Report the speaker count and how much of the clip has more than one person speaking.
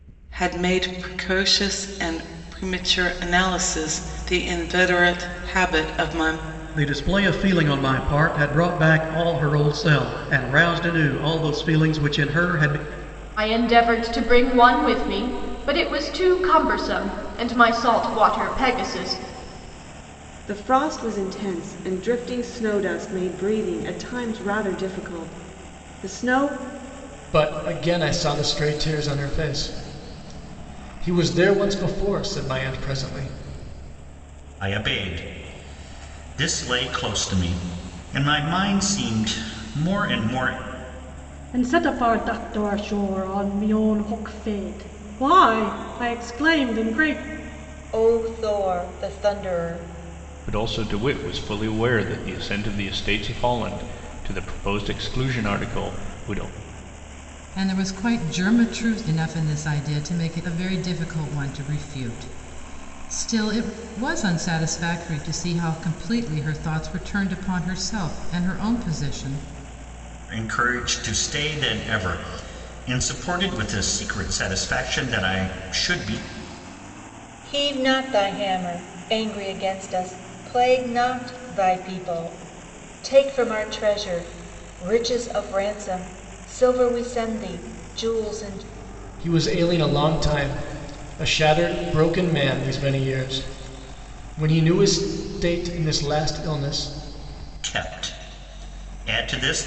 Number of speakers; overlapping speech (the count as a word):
ten, no overlap